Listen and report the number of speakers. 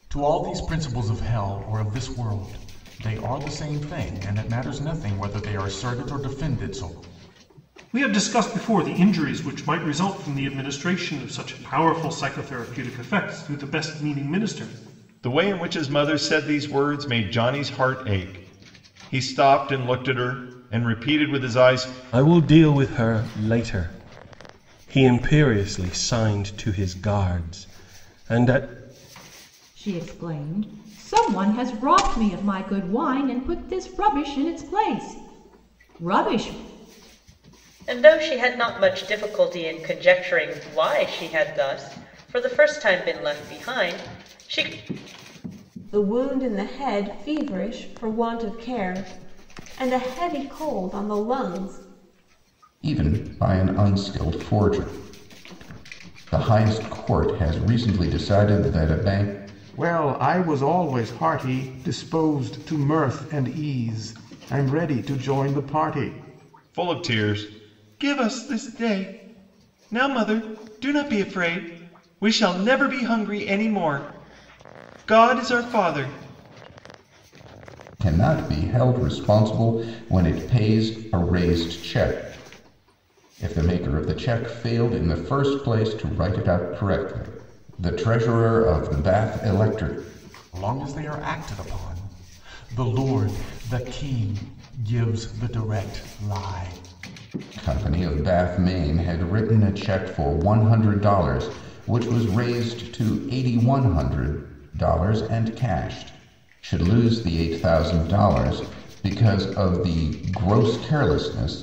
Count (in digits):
9